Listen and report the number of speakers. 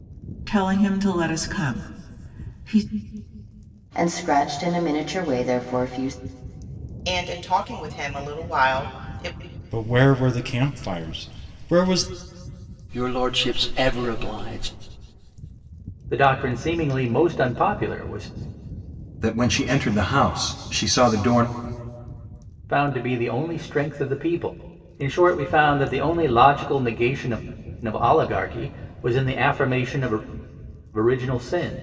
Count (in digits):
7